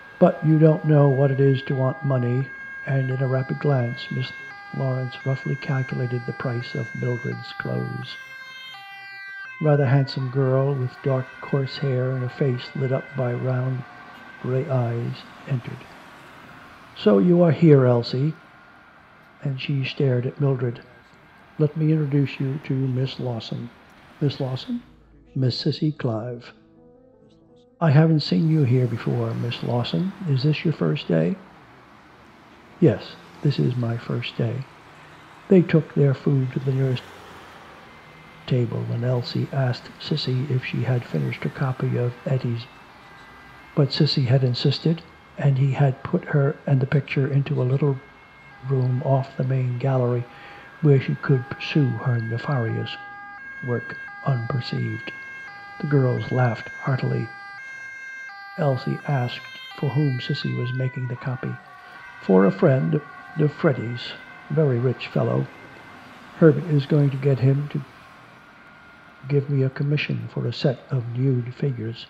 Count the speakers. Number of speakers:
1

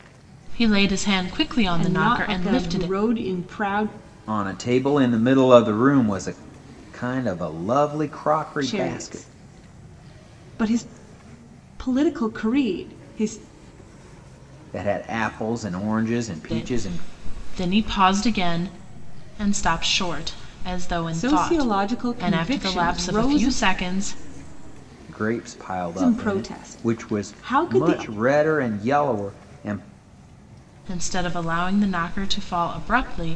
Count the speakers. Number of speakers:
3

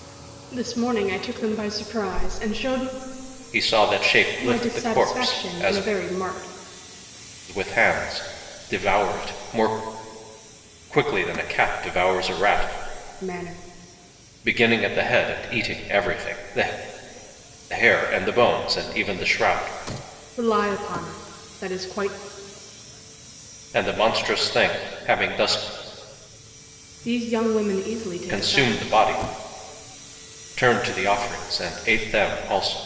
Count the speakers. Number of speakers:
2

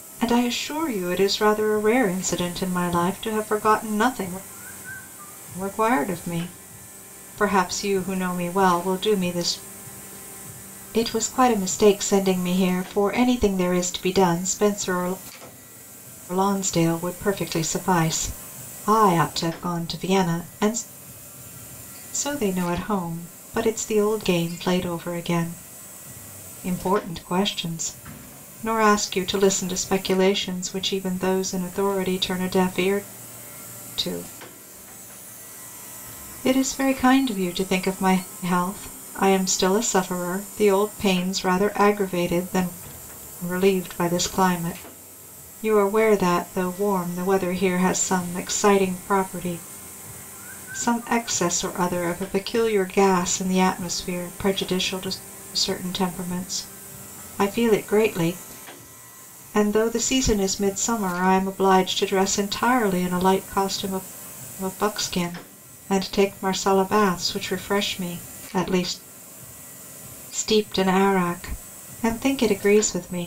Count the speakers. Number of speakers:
1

